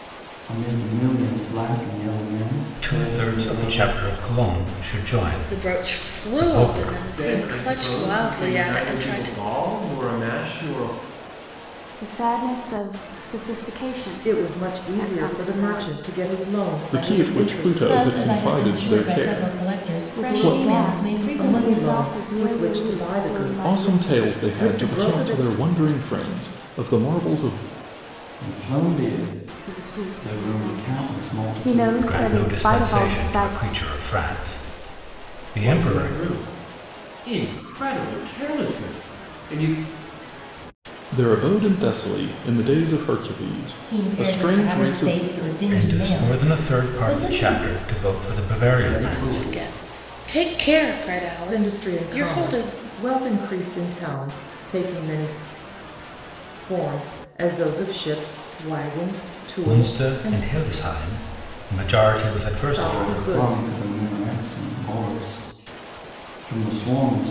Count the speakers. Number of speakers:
8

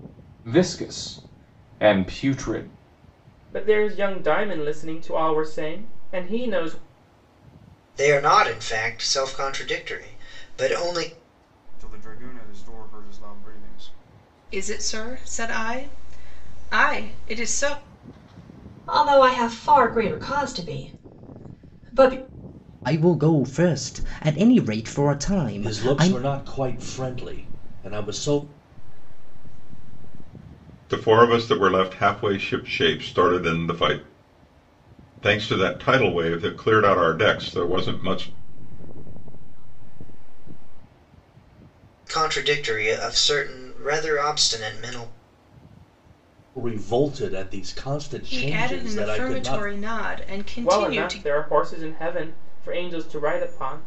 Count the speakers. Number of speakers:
10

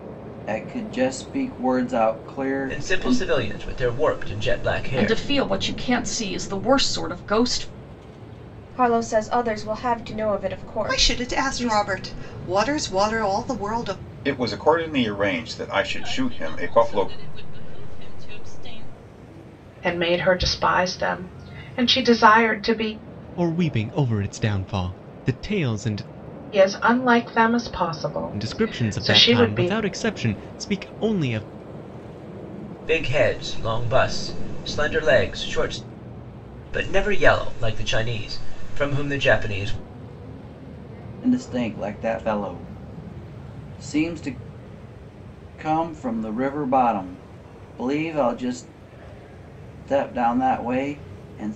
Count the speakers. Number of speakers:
9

